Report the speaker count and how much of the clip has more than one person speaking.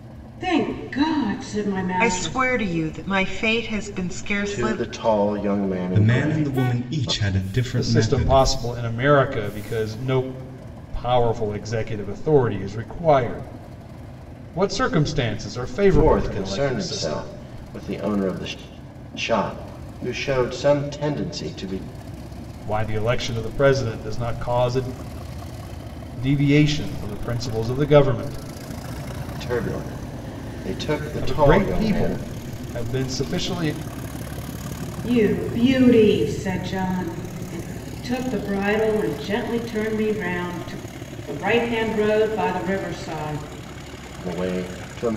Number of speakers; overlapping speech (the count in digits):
5, about 12%